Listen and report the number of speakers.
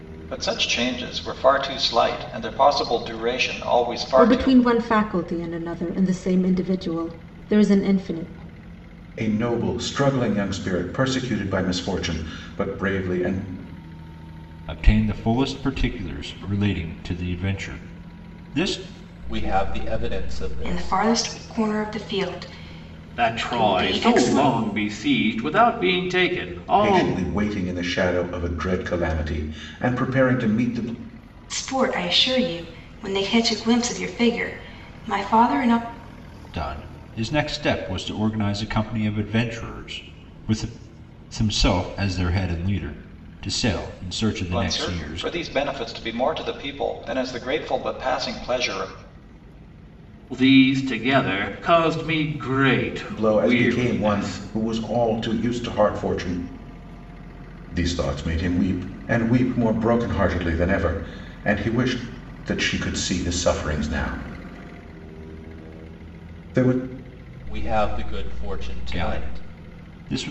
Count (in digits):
7